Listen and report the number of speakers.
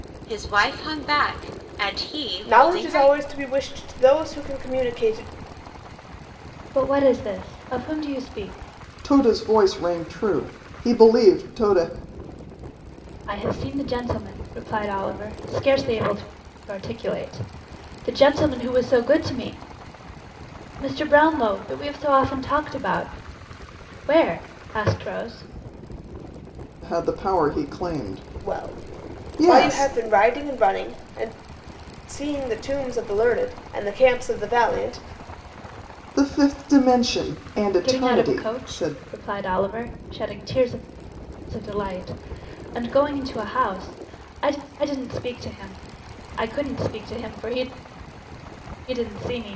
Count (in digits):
4